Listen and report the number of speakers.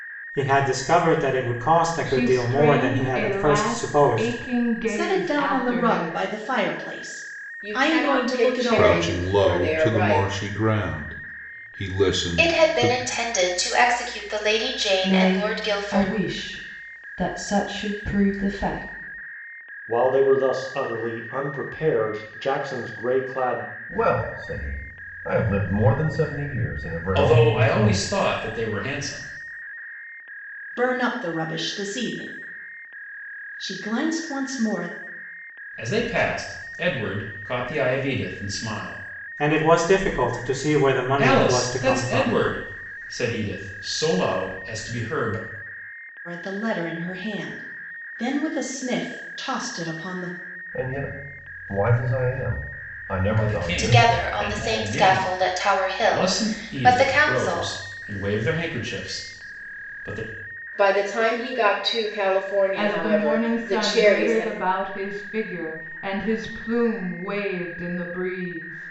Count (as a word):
ten